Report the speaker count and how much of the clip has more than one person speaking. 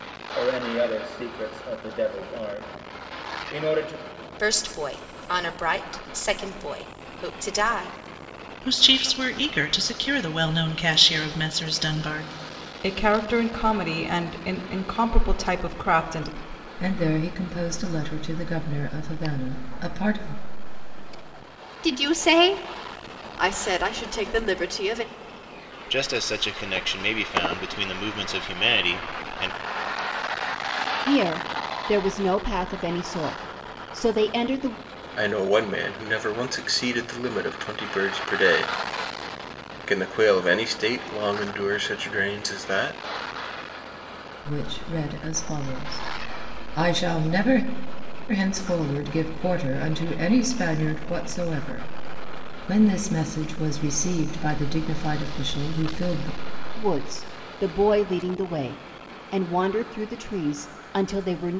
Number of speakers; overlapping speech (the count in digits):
9, no overlap